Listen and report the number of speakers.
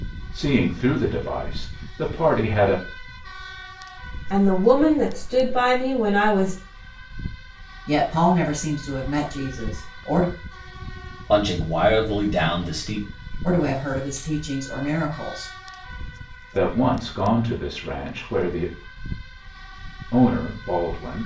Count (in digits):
4